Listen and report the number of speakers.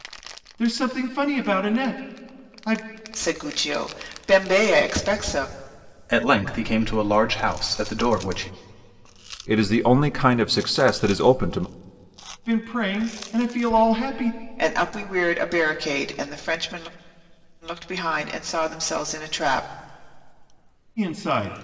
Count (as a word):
four